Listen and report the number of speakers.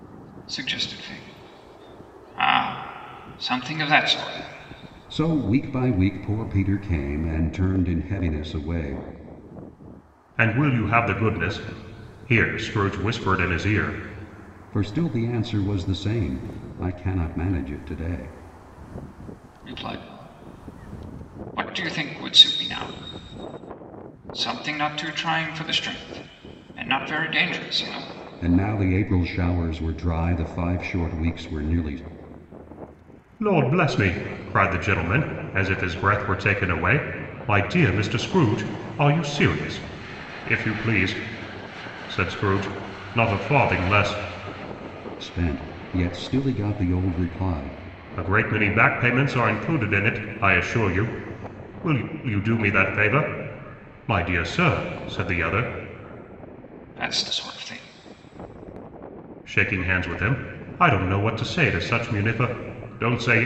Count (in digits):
3